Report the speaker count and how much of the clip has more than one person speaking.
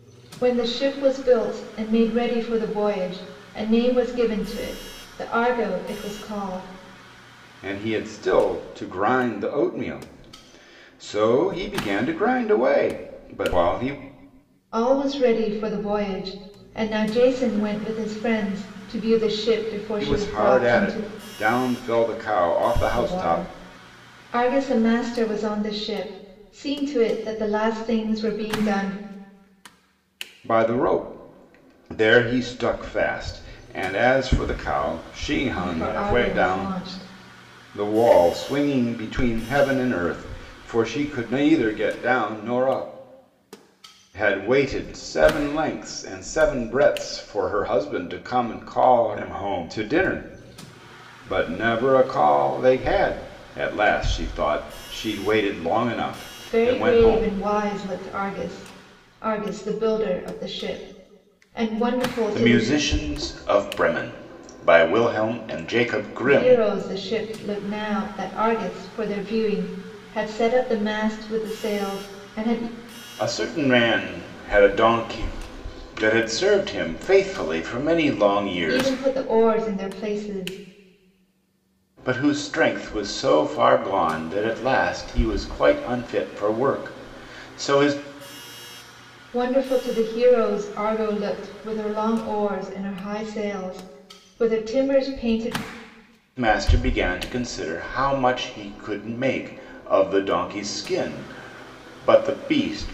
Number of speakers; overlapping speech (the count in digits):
2, about 5%